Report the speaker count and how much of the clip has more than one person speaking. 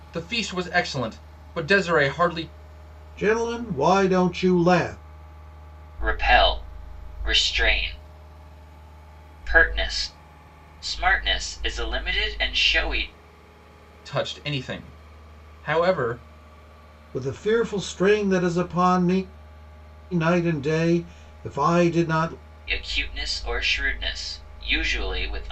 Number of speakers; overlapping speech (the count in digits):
3, no overlap